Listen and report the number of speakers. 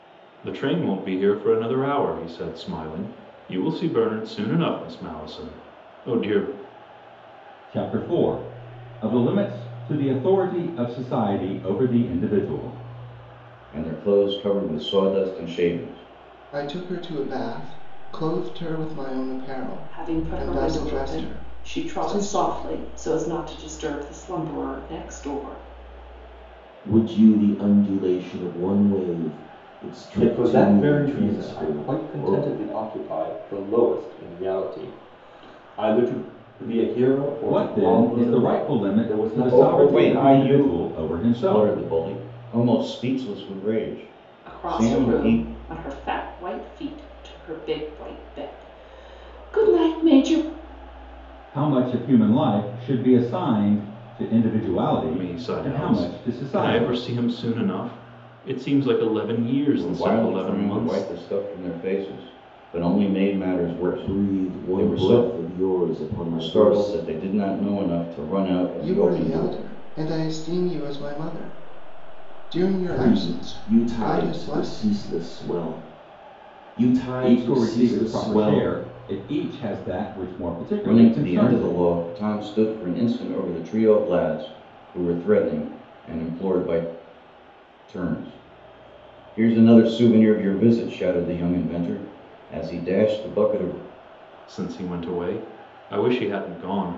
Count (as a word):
seven